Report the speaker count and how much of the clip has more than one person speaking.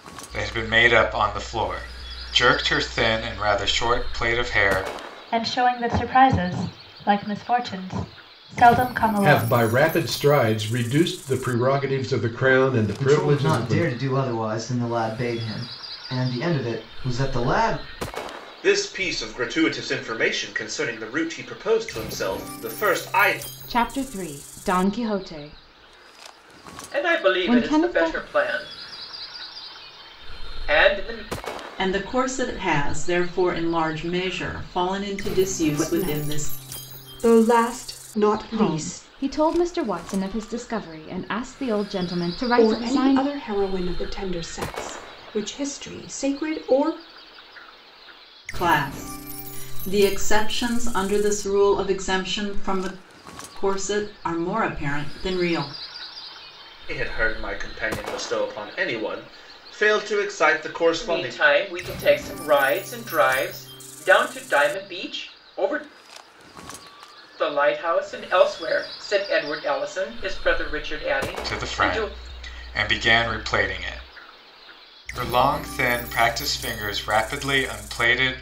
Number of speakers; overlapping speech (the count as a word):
nine, about 8%